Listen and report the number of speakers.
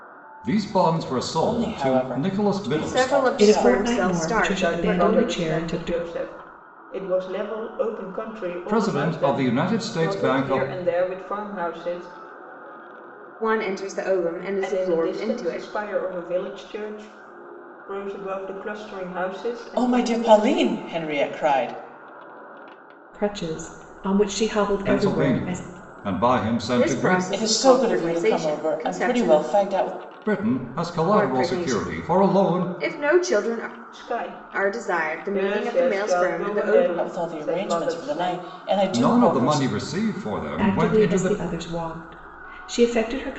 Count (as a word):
five